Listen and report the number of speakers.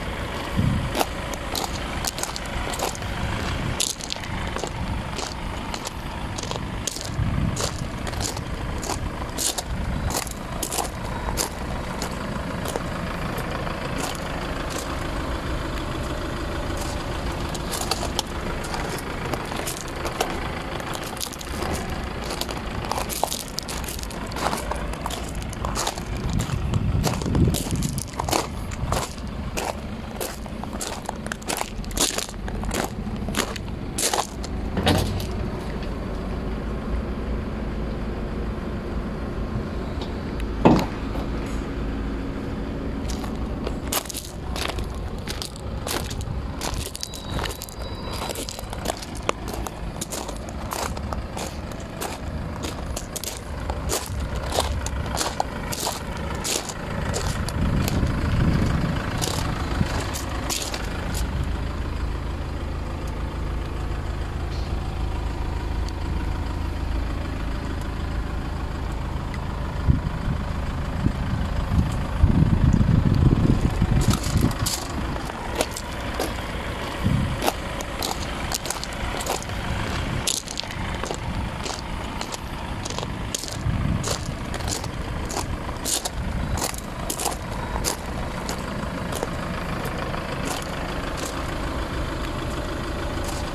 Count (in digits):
0